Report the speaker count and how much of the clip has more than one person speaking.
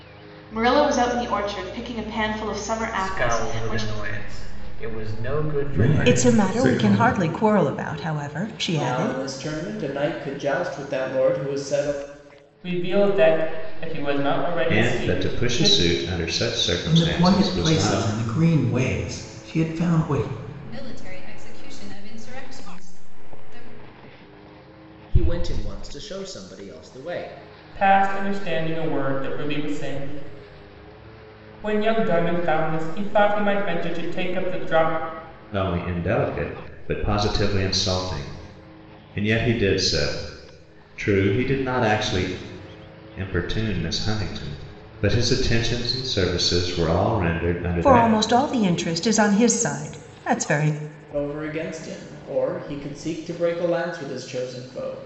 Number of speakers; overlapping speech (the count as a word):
ten, about 10%